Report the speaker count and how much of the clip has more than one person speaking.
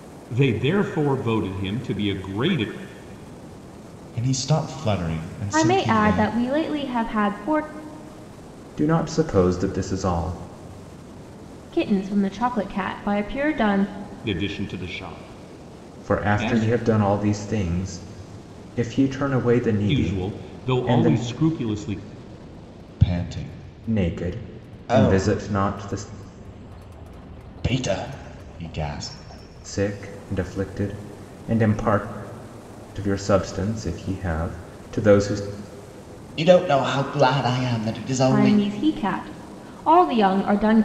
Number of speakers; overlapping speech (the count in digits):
4, about 11%